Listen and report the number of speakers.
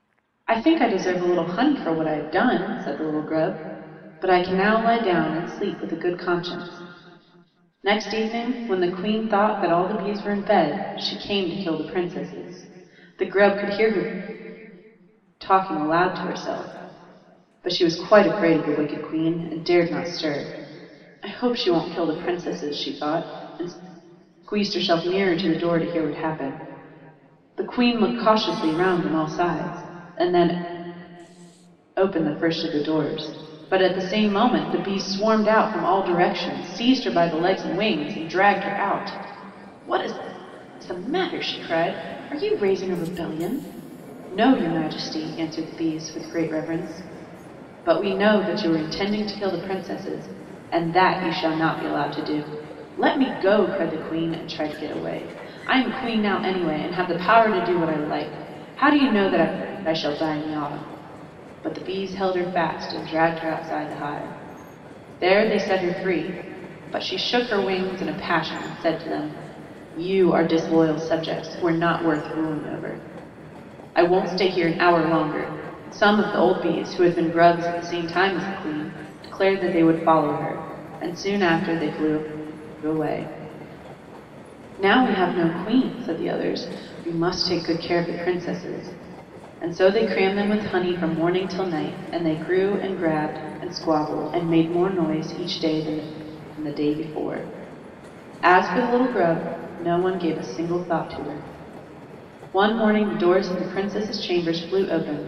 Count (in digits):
1